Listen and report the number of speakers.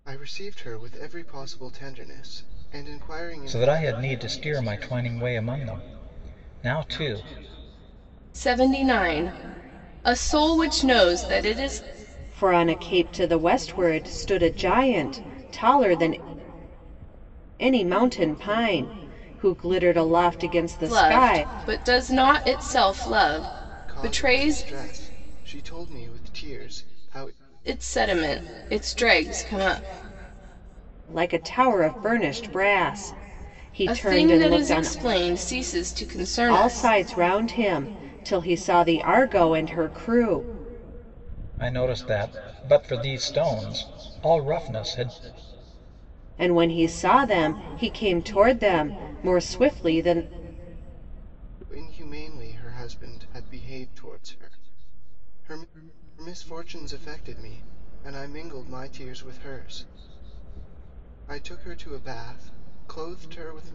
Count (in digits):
4